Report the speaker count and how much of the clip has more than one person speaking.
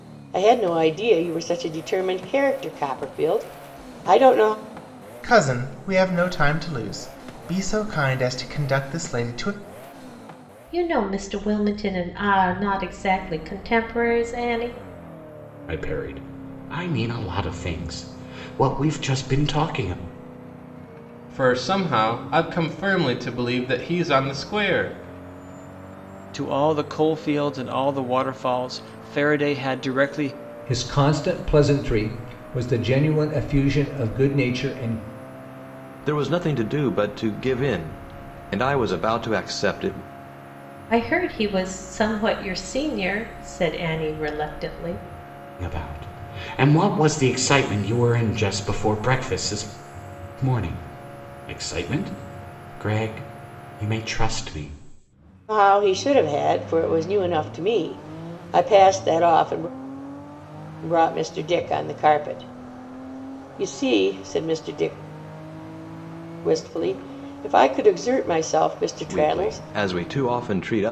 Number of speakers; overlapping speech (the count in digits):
8, about 1%